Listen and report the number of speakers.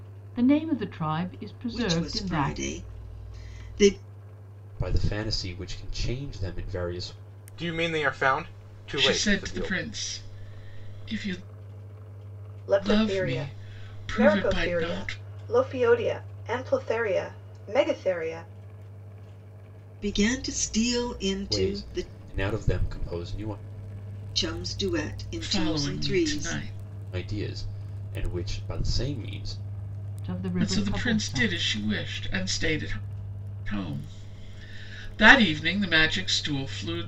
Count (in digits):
6